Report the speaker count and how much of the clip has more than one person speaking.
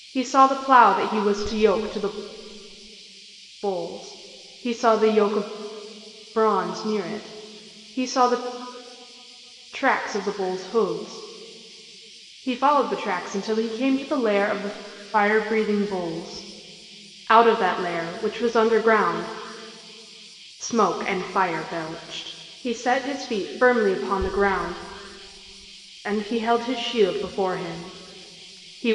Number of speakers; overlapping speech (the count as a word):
one, no overlap